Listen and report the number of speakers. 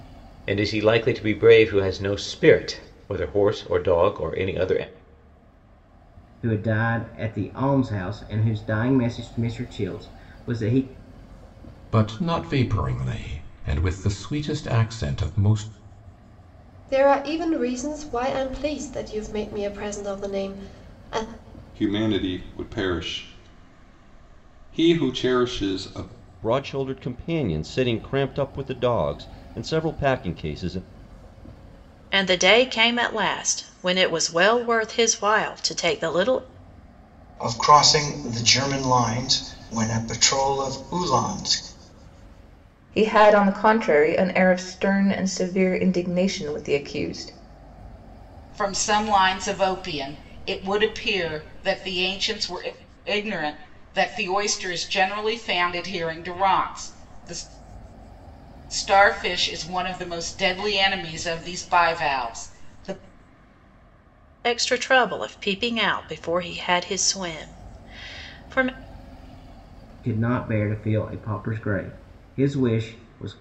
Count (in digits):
10